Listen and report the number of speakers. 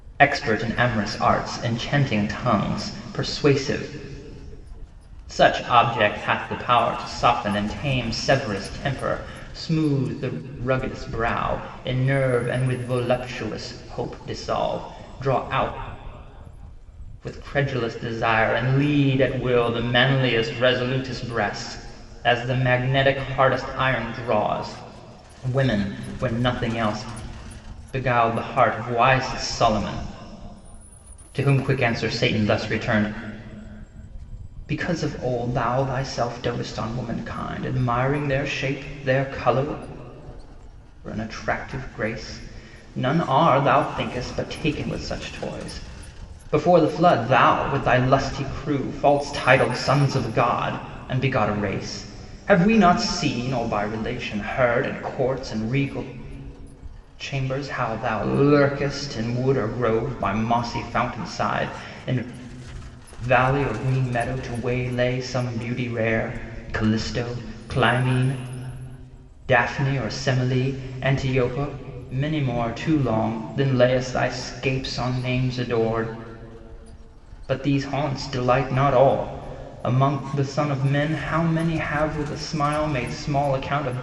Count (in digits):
1